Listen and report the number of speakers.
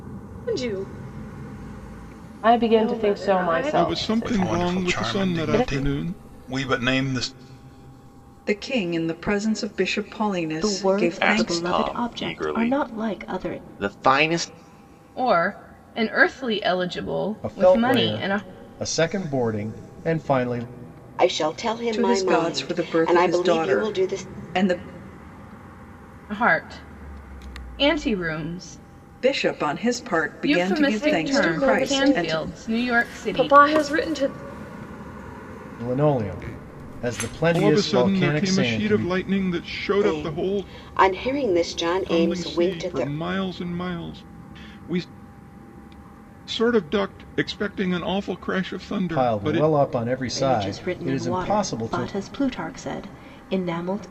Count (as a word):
ten